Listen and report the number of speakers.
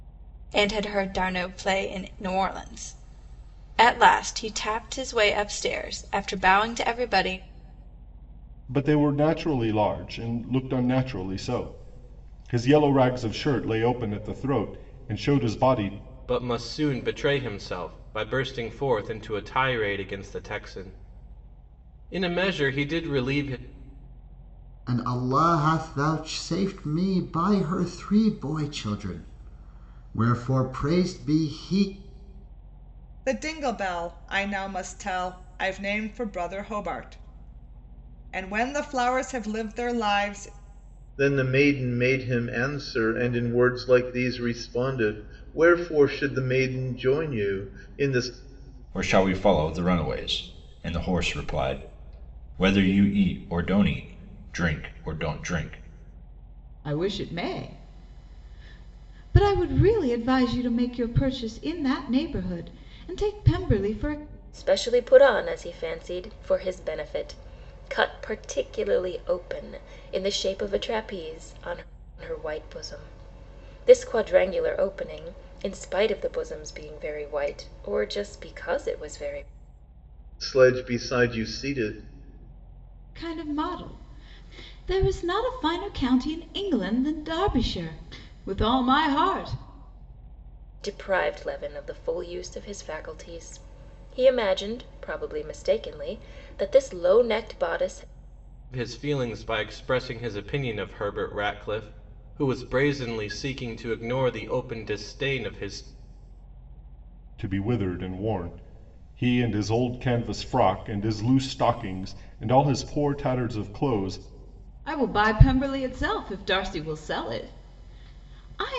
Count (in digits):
9